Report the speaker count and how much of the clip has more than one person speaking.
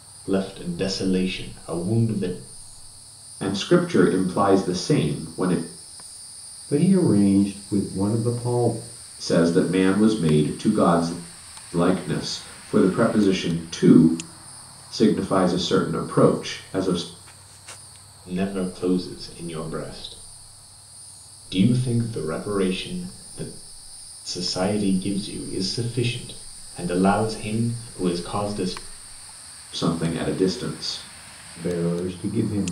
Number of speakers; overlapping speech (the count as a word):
three, no overlap